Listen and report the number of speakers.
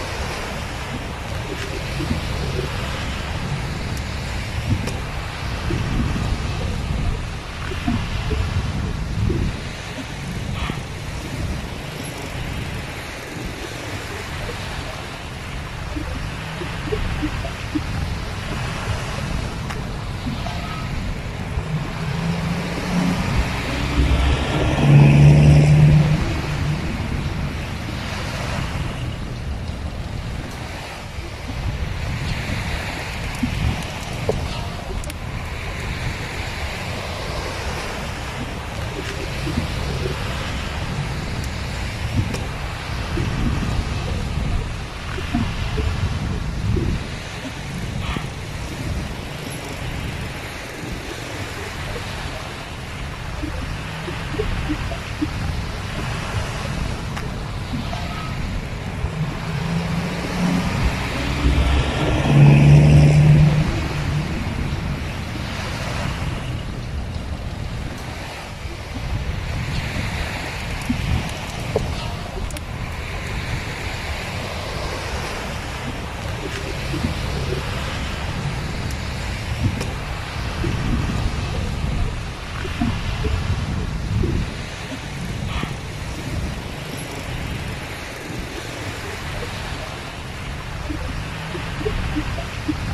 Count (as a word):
zero